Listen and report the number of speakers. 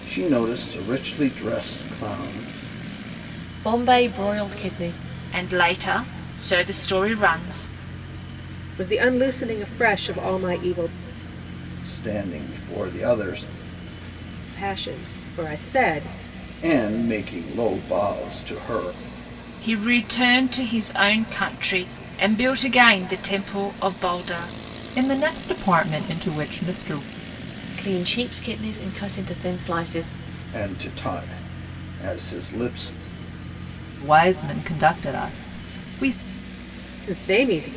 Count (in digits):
4